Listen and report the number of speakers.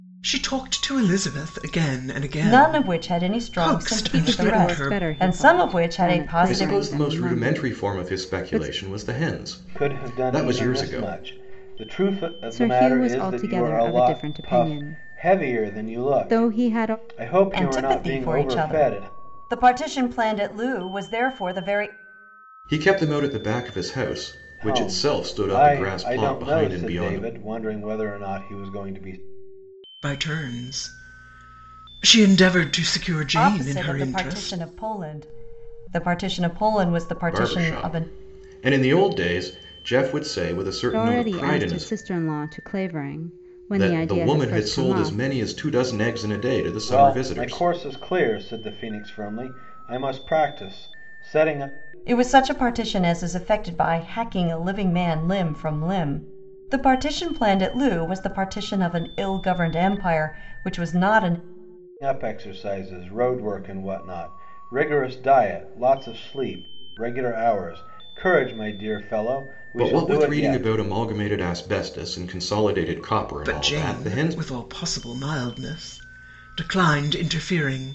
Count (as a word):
five